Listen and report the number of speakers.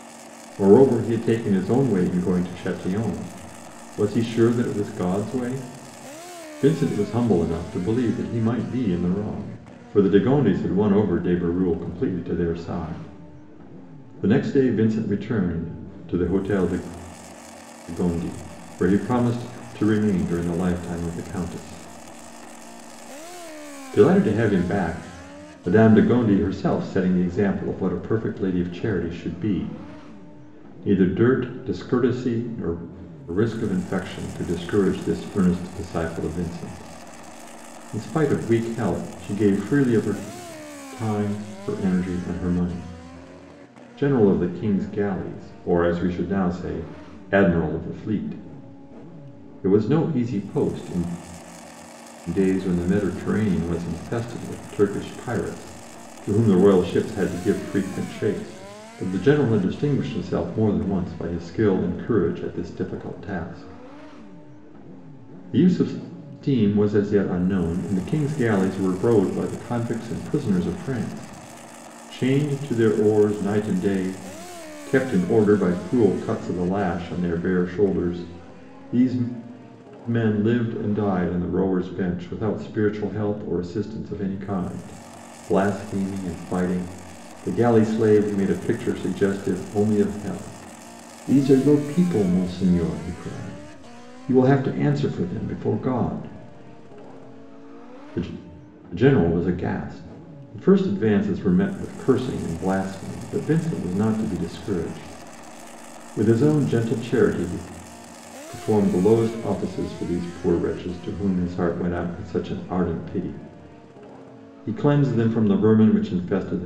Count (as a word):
one